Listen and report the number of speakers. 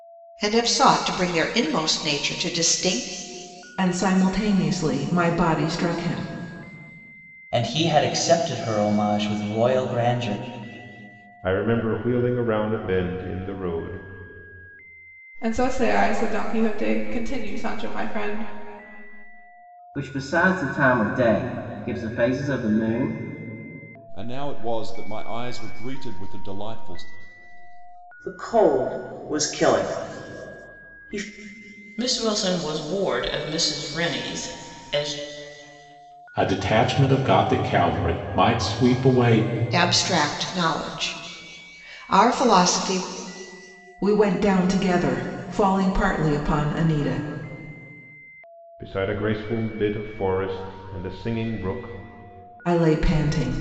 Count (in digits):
10